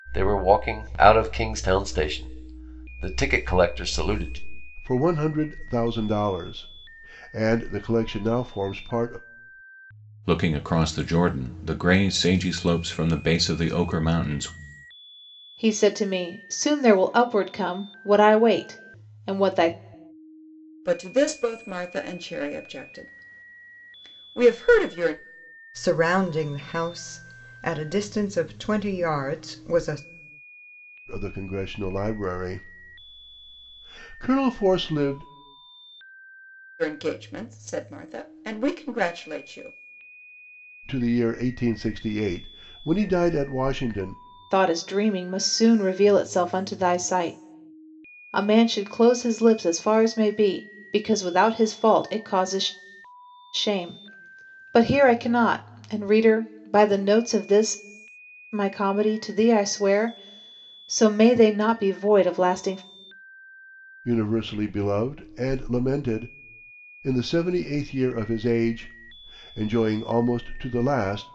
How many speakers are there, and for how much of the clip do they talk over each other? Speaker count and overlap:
6, no overlap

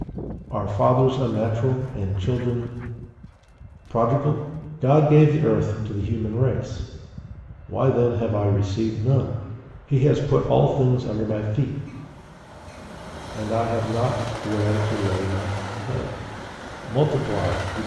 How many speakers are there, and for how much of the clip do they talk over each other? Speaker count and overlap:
1, no overlap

